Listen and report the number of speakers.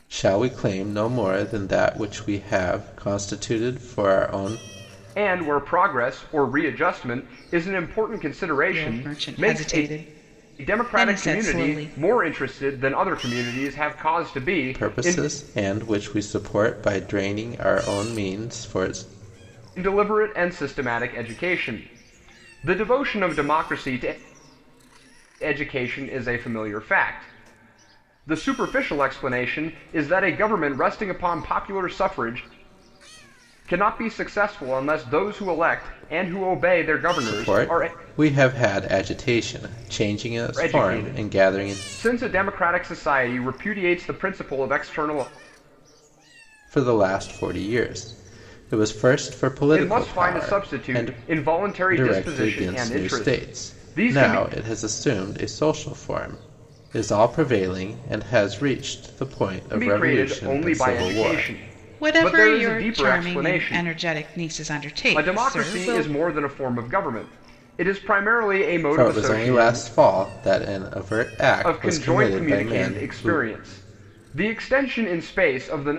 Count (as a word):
three